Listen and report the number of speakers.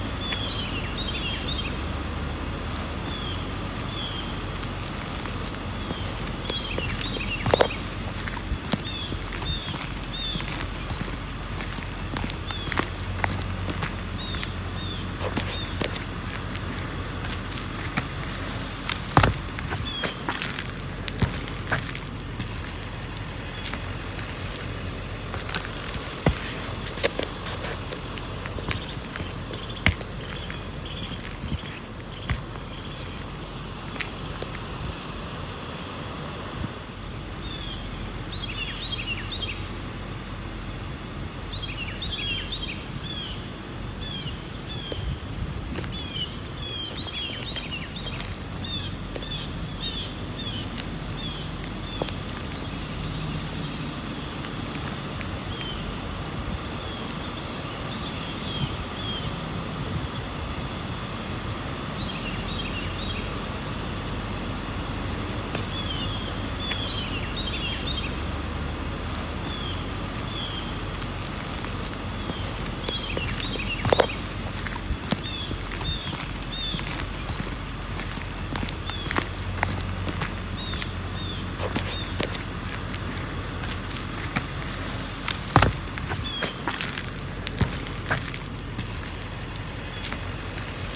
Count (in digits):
0